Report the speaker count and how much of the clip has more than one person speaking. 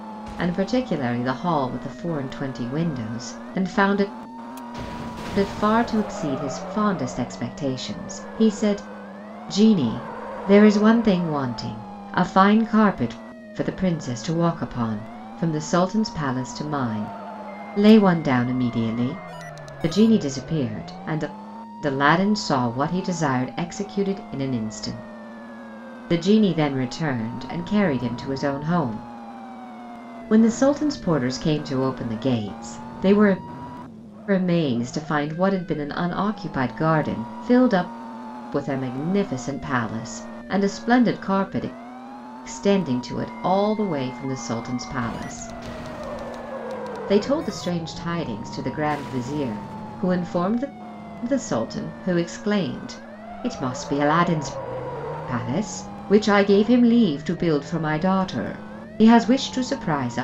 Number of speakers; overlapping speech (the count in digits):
1, no overlap